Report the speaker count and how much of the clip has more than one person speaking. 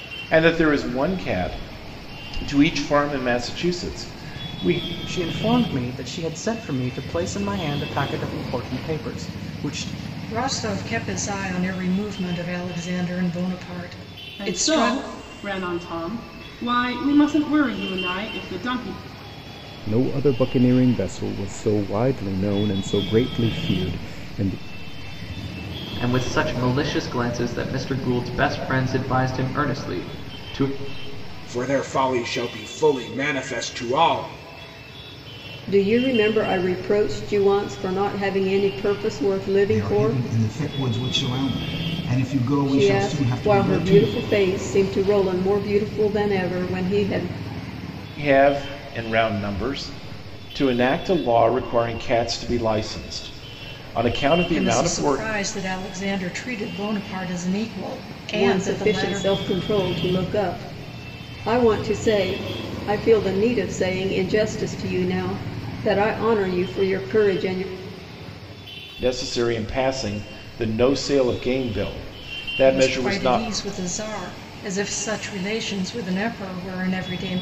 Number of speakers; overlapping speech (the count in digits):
9, about 7%